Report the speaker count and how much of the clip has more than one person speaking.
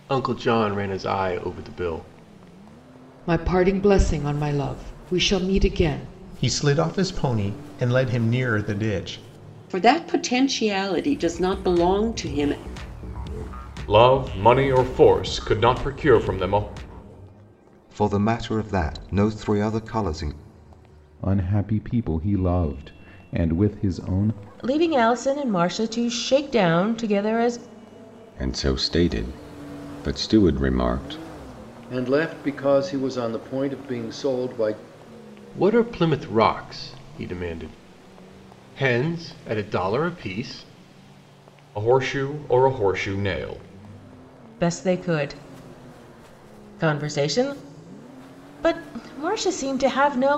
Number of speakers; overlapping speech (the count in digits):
10, no overlap